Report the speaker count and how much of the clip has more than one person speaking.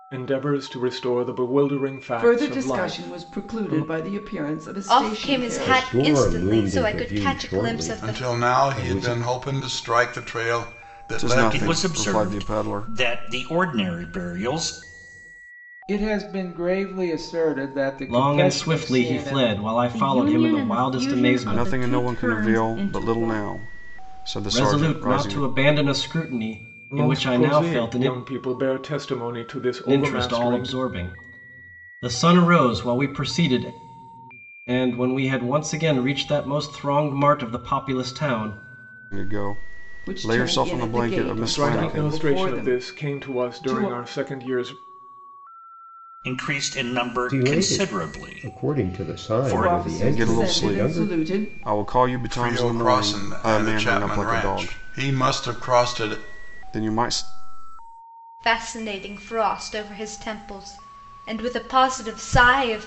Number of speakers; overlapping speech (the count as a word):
ten, about 45%